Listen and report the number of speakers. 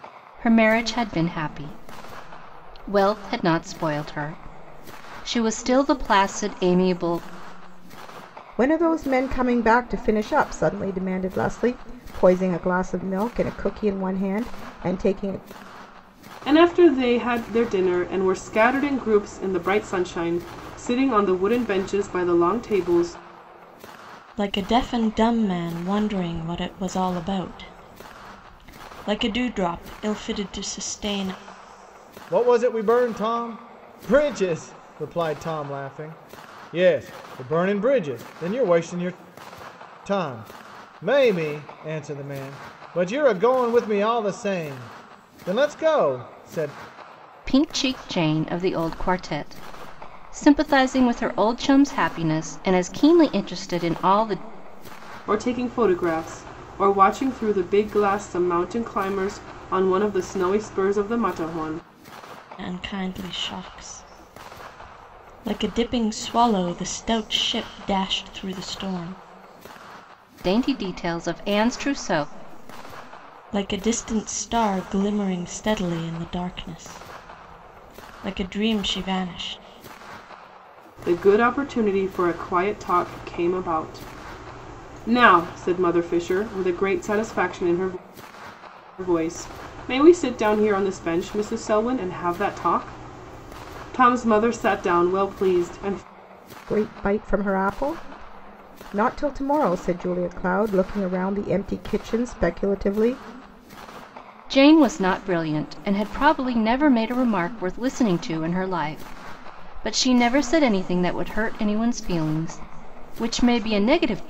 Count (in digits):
5